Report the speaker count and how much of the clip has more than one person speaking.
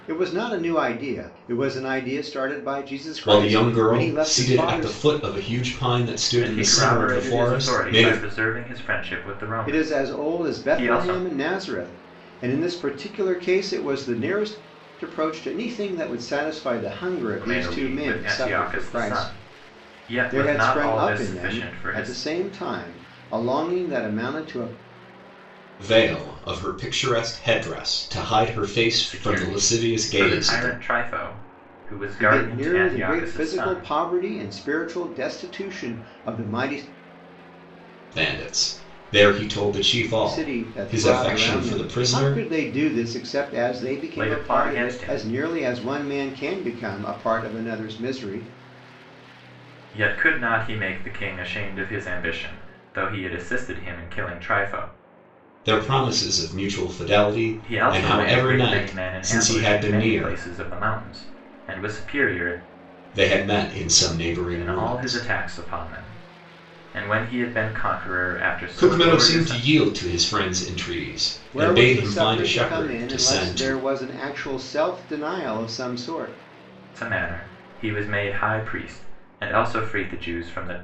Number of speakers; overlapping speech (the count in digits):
3, about 28%